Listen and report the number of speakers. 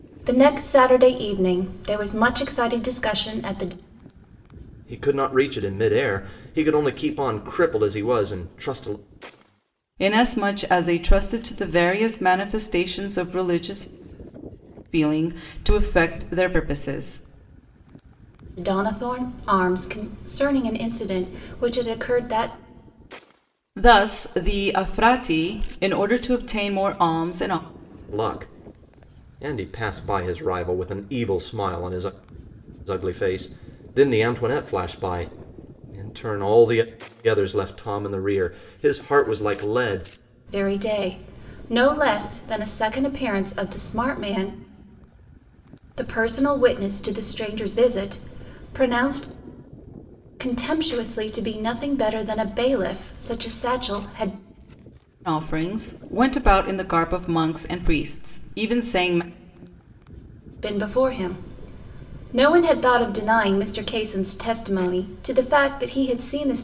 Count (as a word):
three